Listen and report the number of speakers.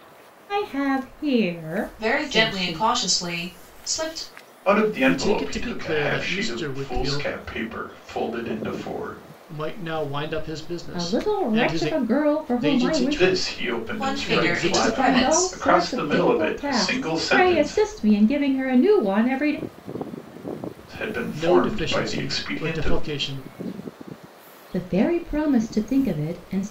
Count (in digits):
4